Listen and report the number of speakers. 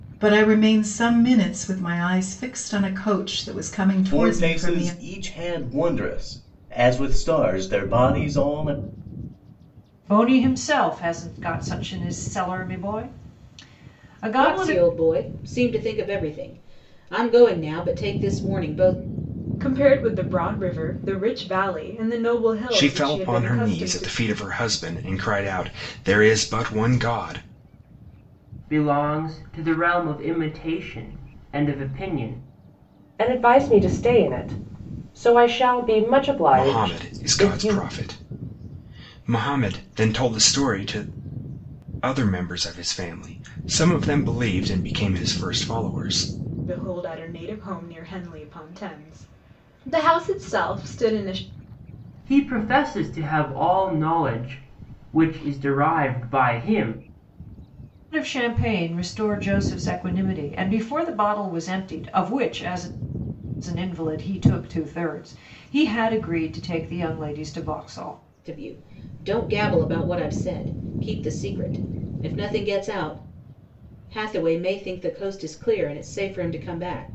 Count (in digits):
8